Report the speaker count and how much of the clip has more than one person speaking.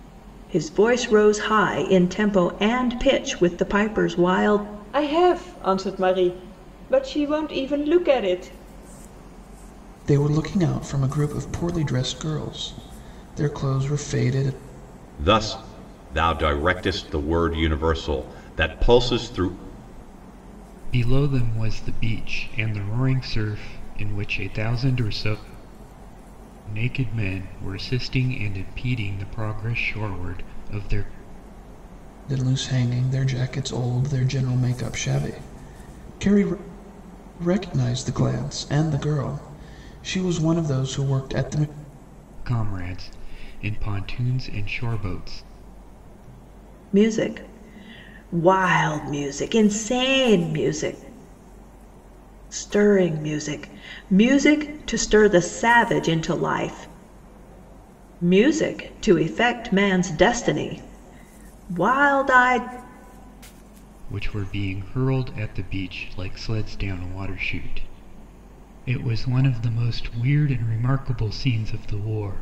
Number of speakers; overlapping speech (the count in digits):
5, no overlap